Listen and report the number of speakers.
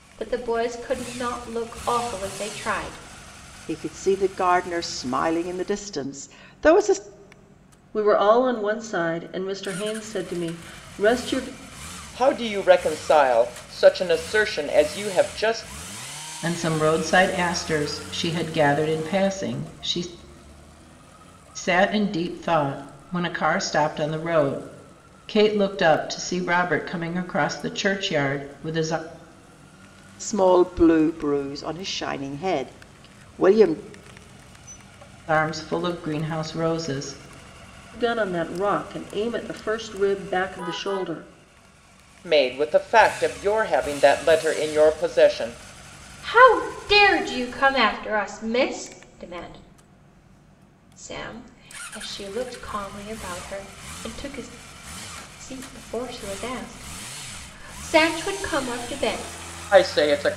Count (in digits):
5